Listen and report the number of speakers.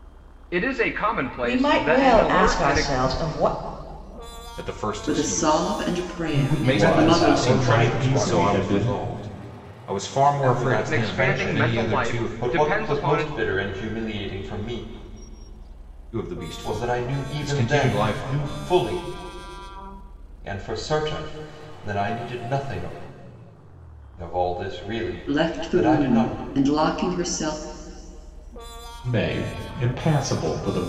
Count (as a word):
six